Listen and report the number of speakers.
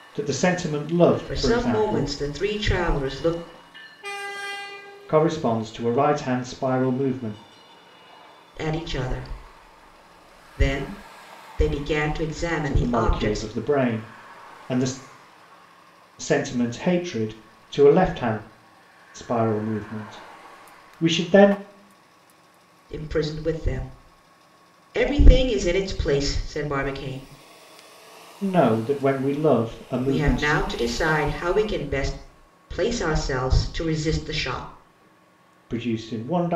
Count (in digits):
2